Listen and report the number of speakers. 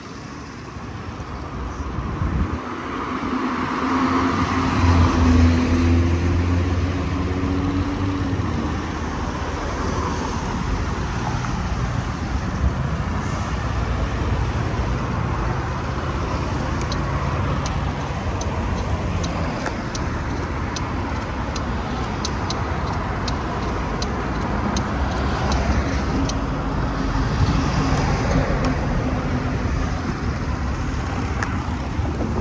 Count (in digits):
0